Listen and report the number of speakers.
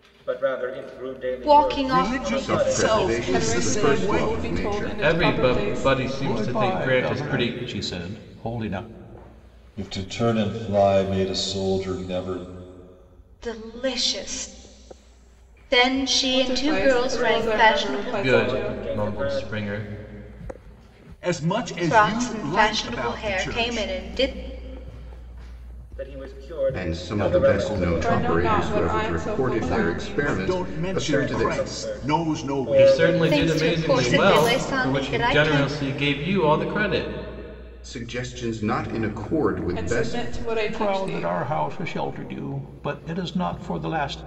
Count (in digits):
8